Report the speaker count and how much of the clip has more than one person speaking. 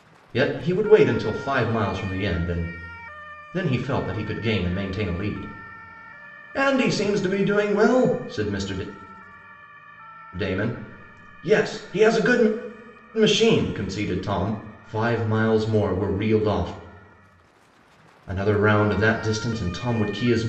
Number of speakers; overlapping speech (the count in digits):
1, no overlap